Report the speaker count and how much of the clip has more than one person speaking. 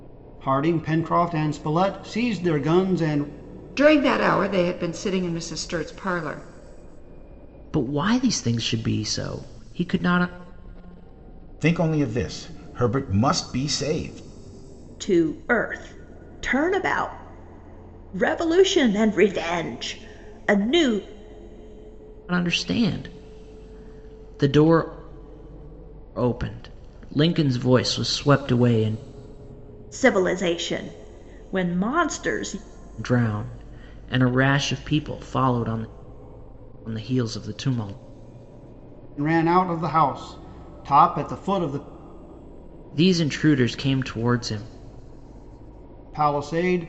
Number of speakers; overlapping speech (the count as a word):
five, no overlap